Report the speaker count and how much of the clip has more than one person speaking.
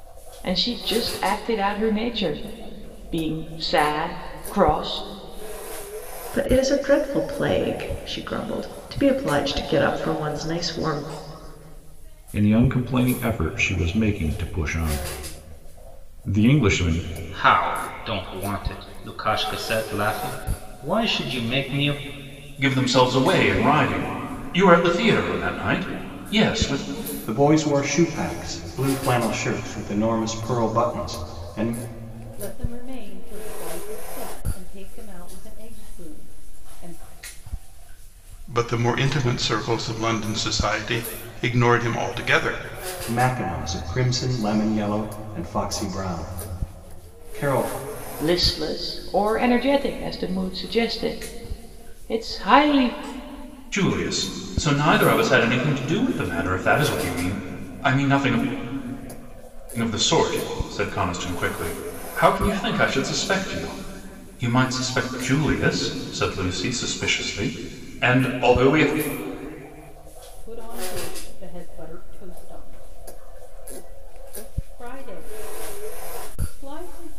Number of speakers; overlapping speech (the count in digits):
8, no overlap